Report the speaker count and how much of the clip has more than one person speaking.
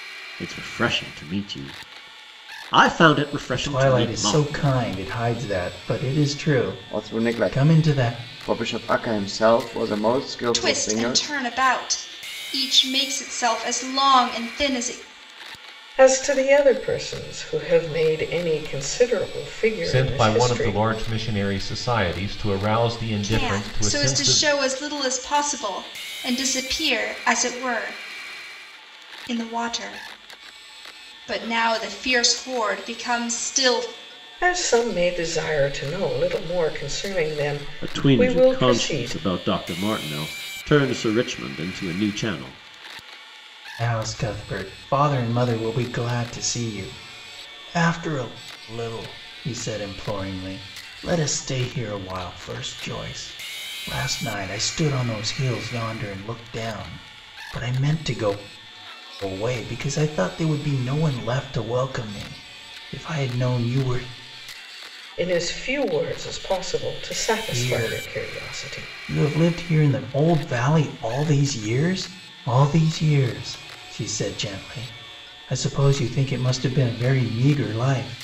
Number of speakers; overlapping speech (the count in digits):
6, about 11%